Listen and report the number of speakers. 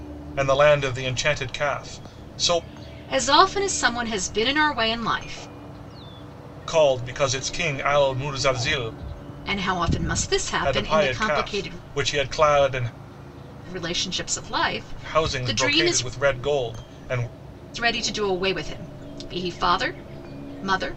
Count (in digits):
2